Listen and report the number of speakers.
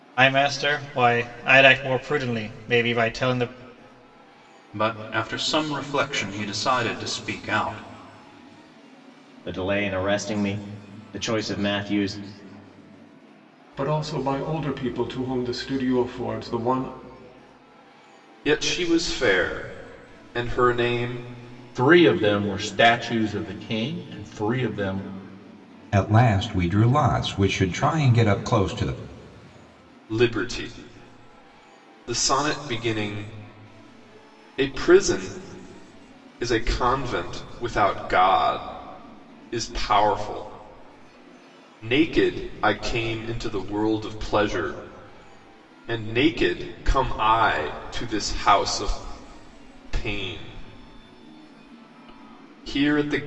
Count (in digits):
7